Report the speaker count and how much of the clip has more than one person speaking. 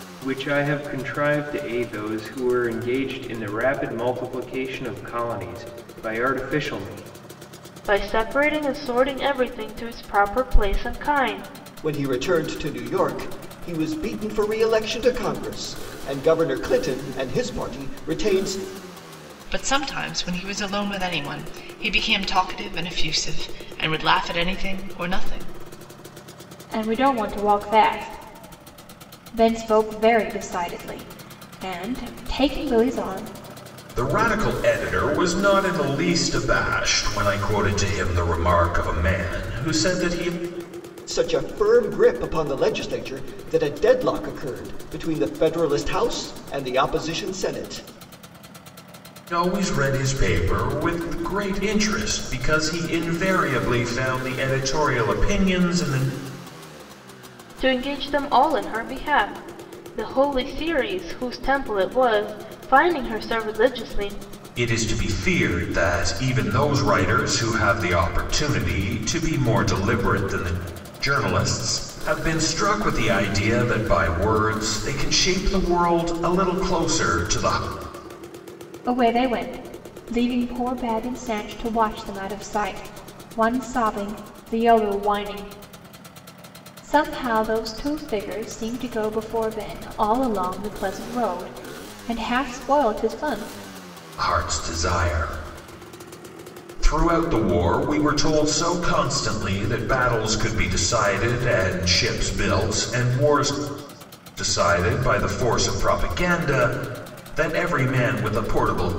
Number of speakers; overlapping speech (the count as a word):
six, no overlap